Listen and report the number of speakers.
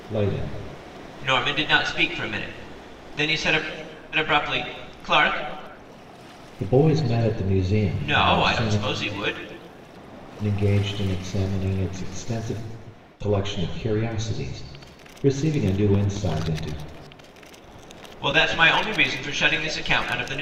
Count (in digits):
2